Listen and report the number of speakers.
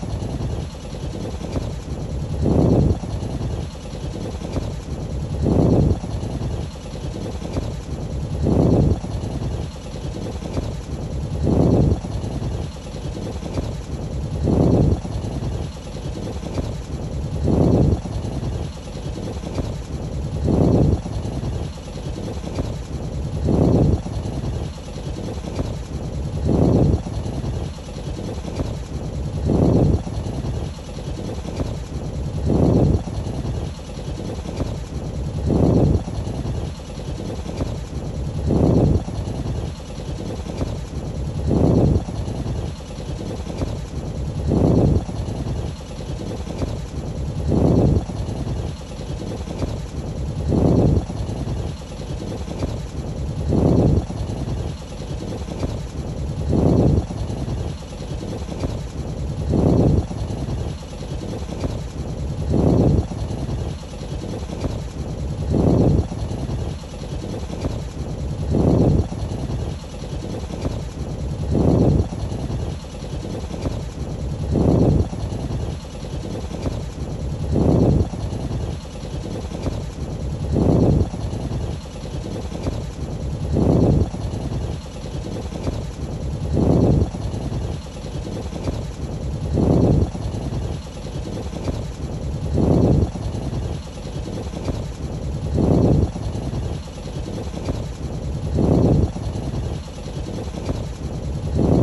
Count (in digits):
0